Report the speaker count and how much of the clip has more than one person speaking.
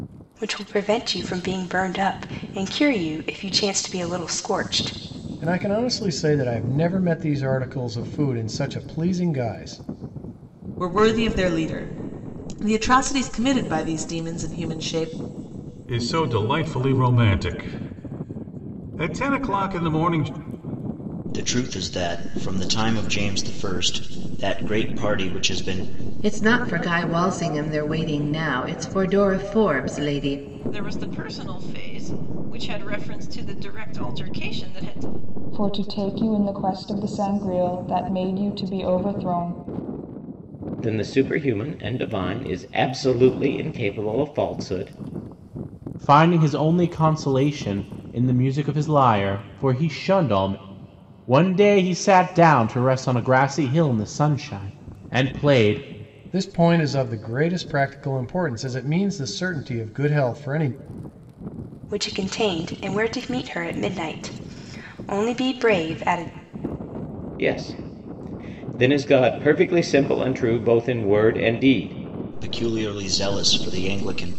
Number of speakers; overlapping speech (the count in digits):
10, no overlap